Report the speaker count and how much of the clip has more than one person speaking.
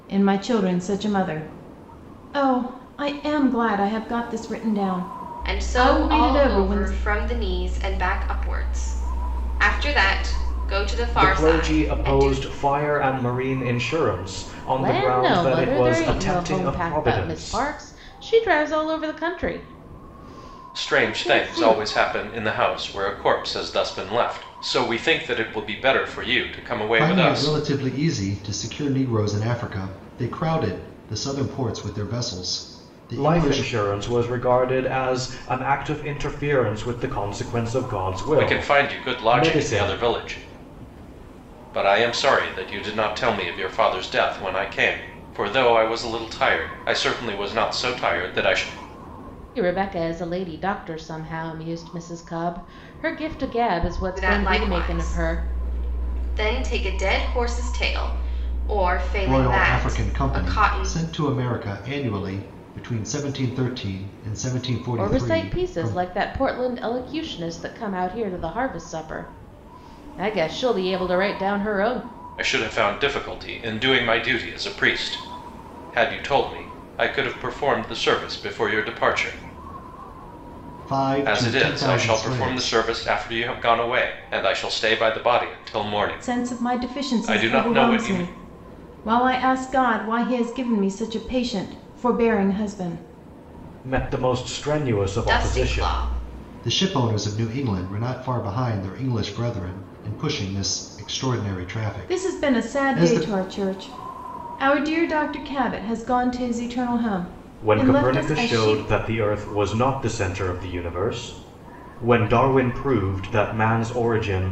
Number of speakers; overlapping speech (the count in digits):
6, about 18%